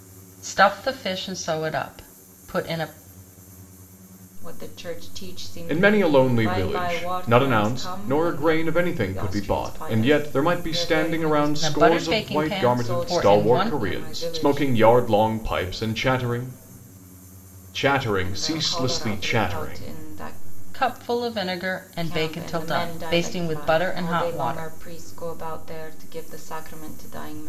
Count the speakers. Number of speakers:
three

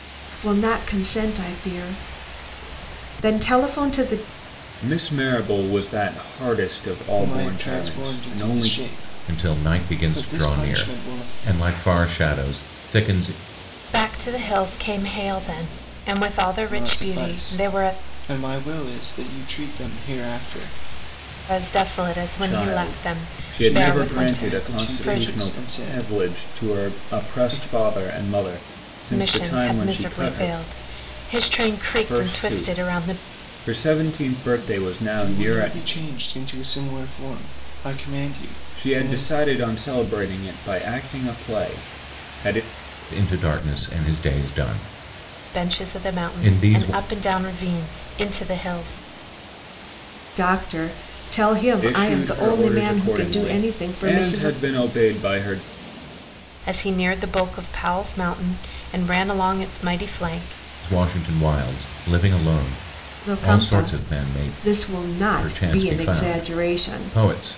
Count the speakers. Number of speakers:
five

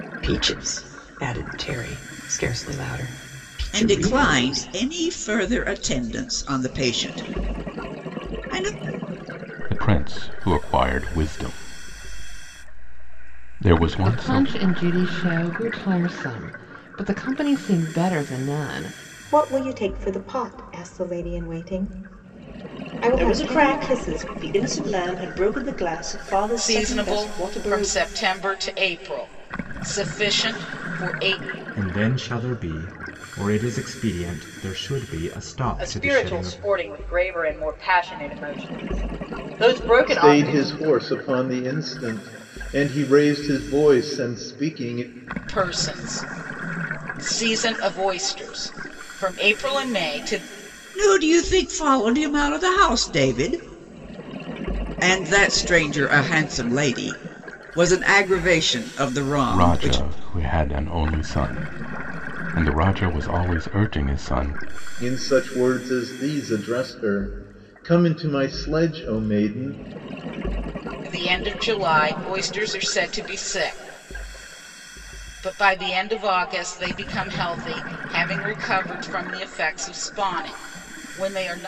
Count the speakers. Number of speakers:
ten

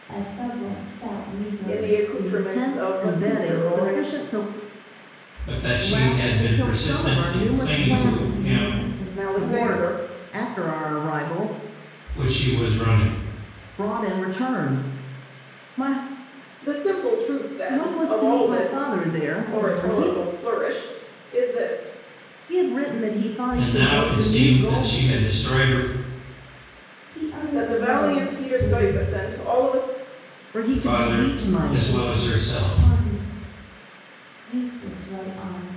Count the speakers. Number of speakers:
four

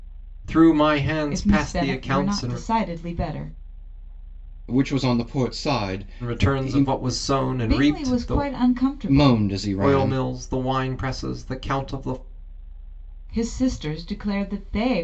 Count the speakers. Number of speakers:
three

